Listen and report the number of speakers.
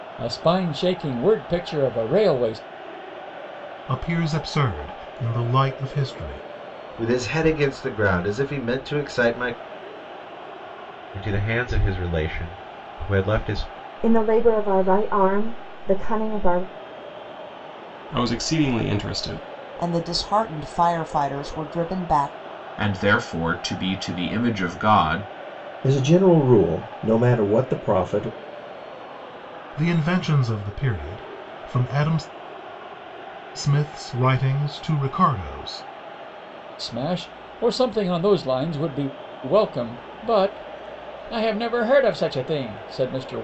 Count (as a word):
nine